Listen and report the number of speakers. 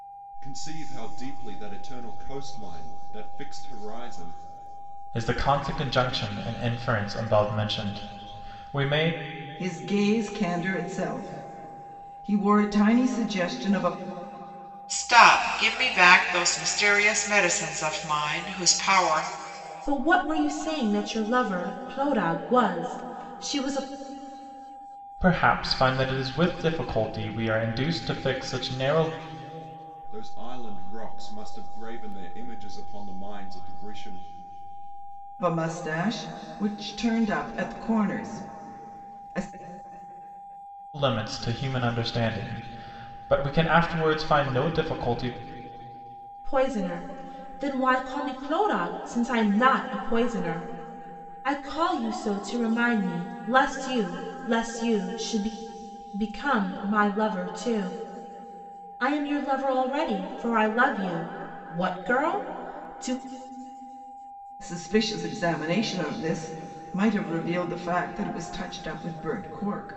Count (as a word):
five